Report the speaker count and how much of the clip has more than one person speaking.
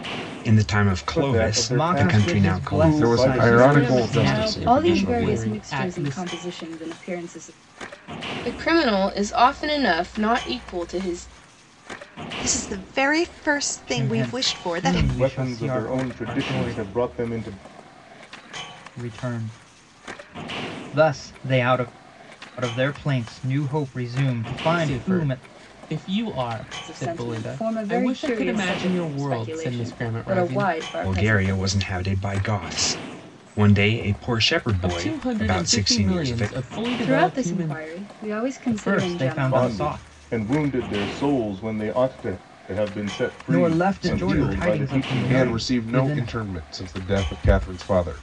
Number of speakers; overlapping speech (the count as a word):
eight, about 42%